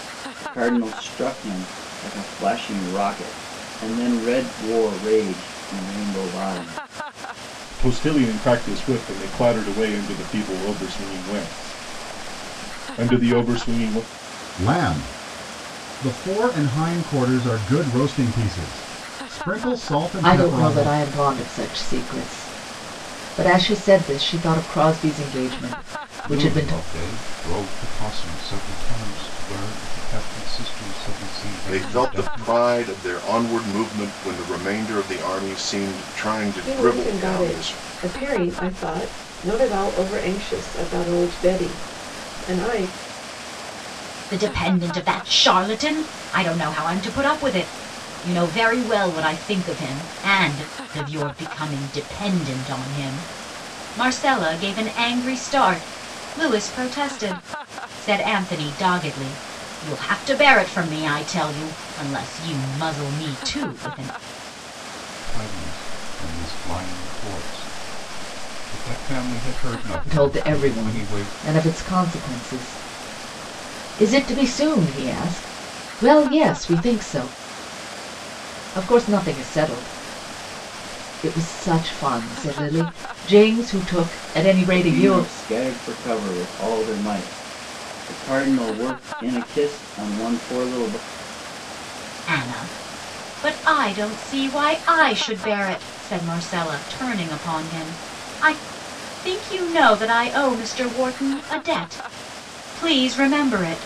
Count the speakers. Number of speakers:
8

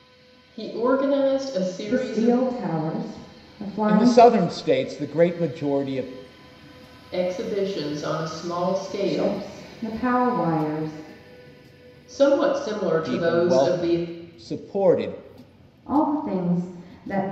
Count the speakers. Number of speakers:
3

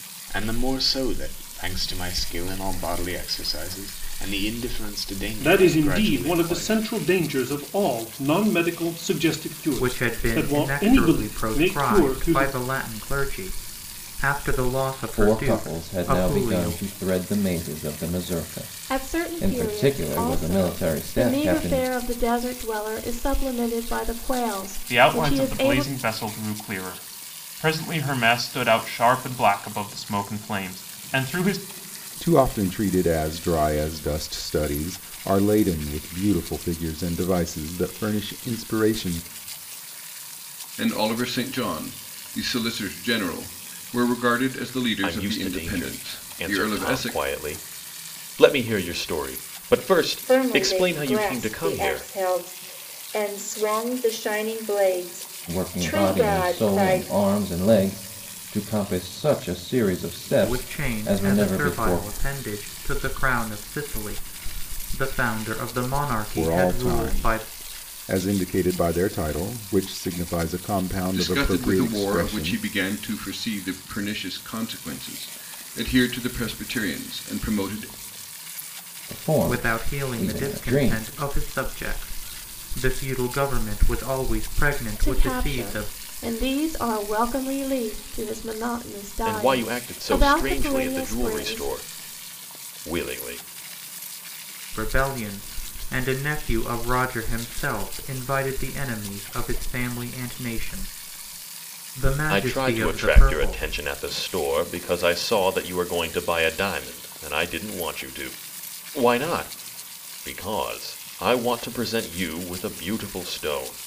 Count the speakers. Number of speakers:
10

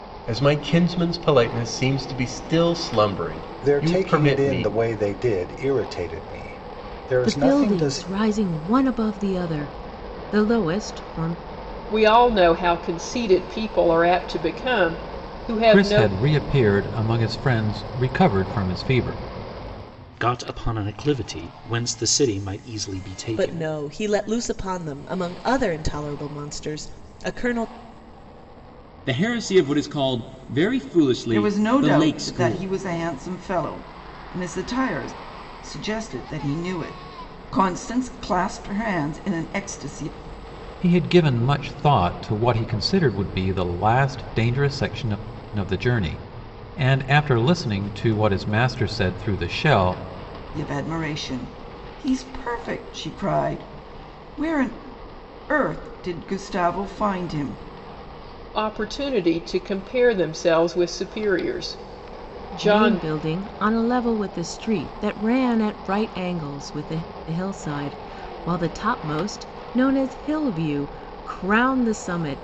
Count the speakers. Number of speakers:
9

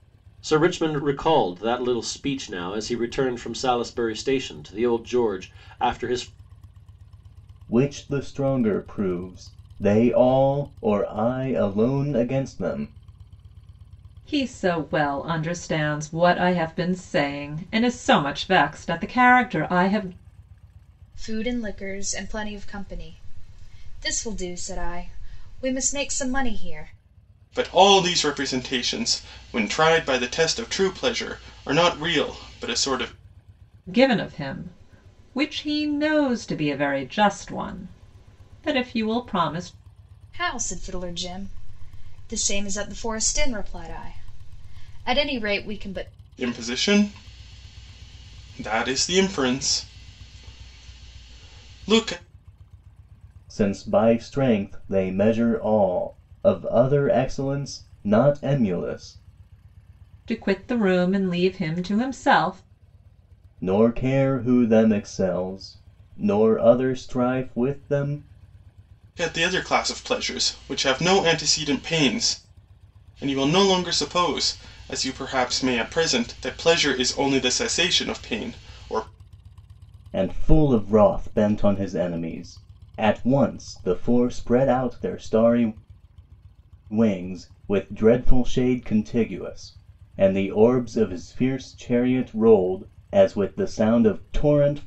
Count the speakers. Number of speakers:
5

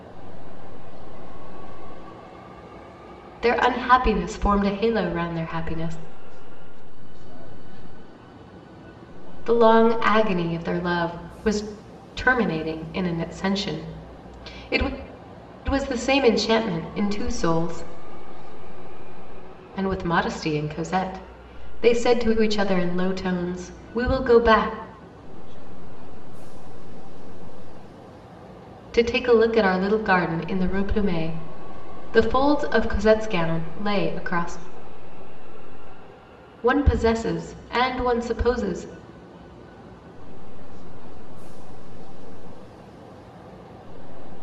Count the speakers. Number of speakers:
2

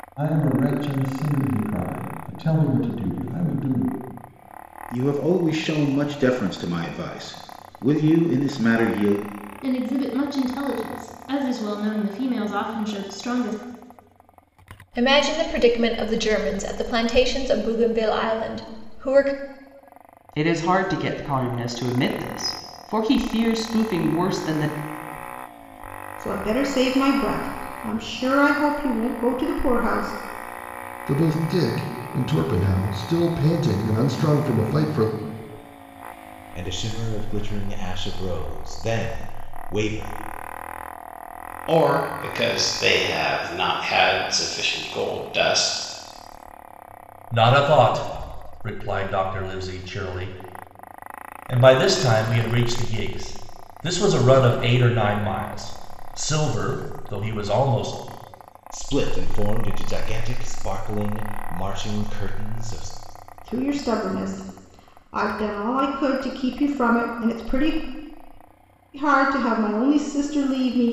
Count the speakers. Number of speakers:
10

